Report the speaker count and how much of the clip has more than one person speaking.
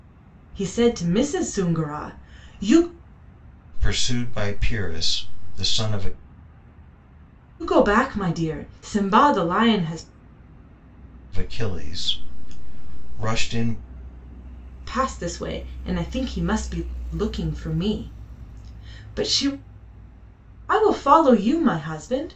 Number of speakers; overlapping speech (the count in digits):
2, no overlap